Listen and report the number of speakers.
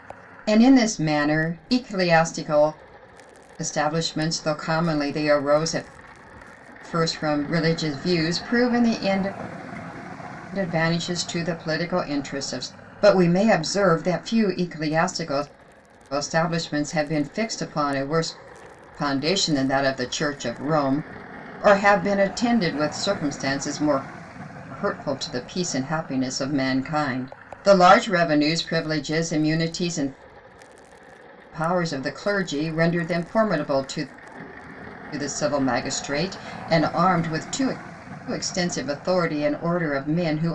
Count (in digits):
1